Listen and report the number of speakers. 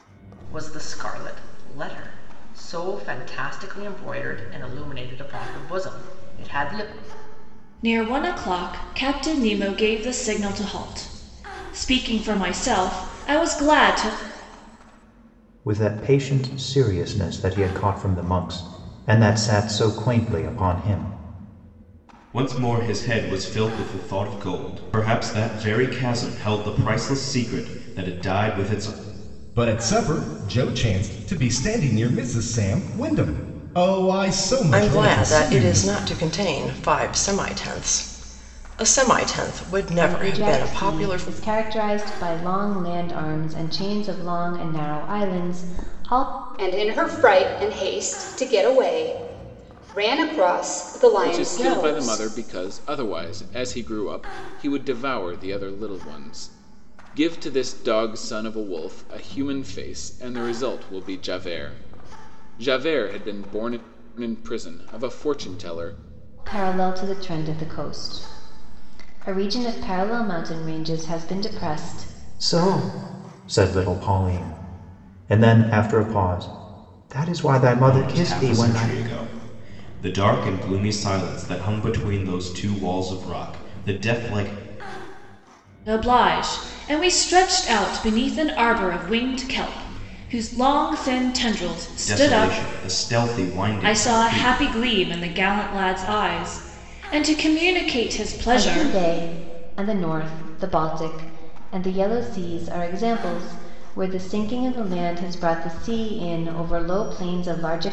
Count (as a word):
nine